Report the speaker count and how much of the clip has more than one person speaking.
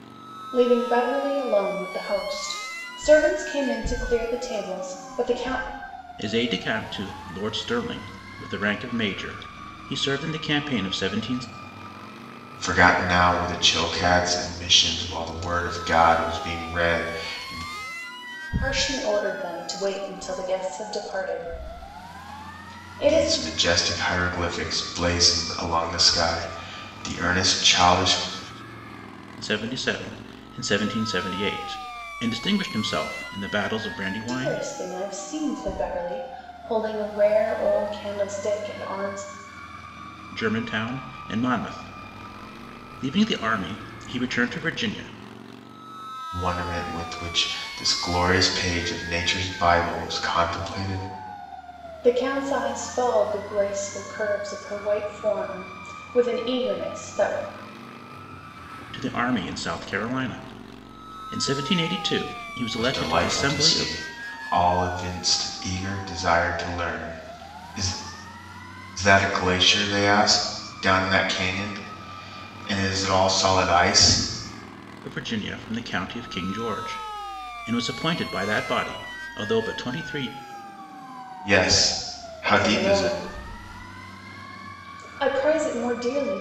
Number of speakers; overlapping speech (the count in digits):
3, about 3%